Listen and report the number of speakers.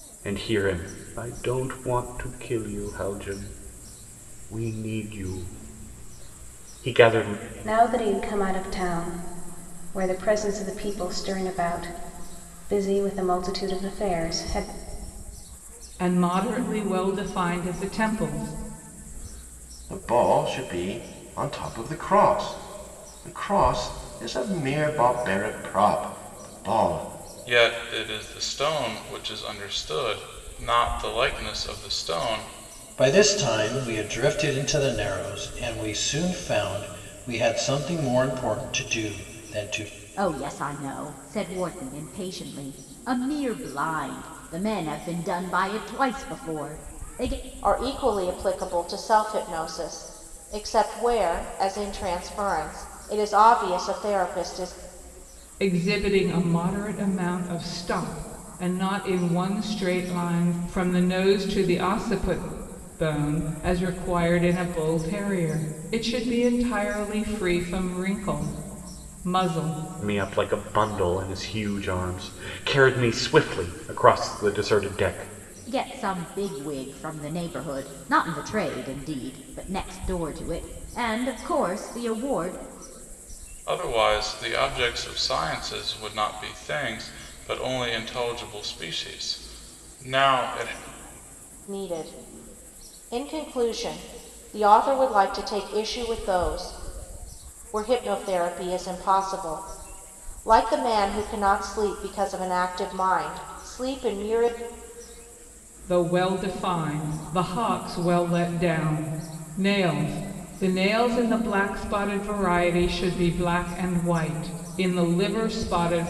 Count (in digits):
8